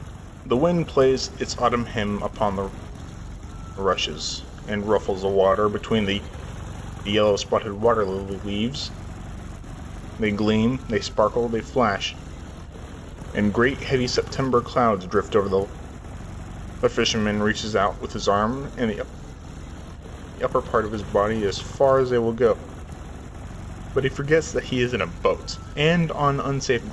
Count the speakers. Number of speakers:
1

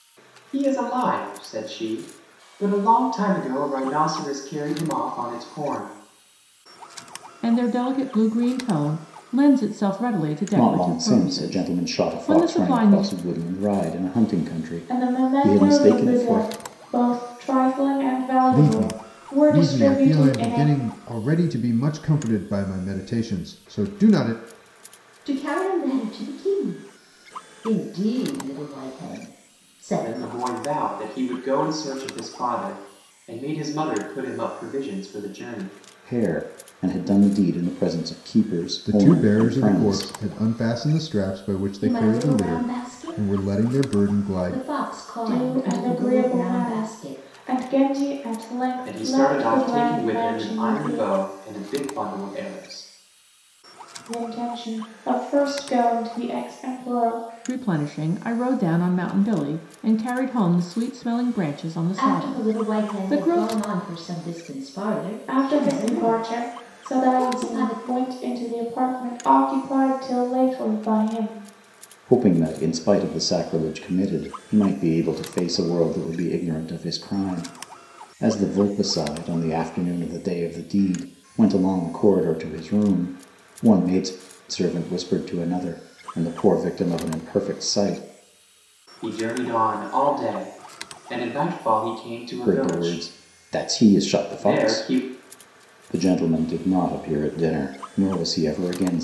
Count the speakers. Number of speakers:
6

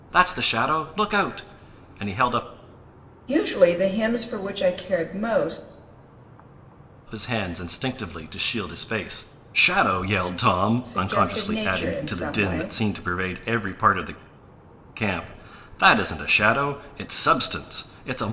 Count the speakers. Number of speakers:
2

